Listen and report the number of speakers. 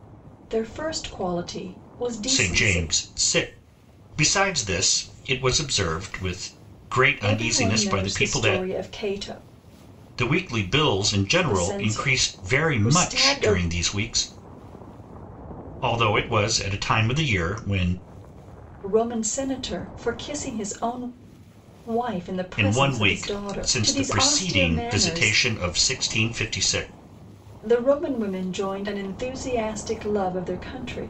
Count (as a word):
two